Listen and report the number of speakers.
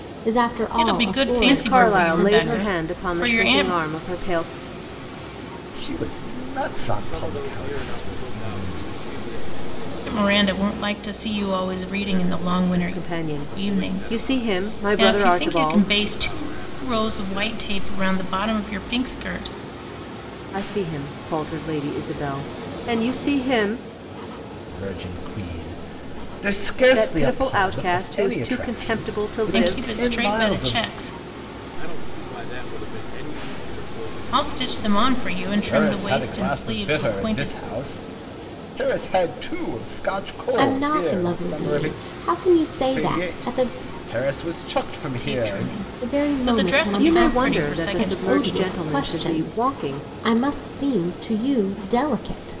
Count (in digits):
5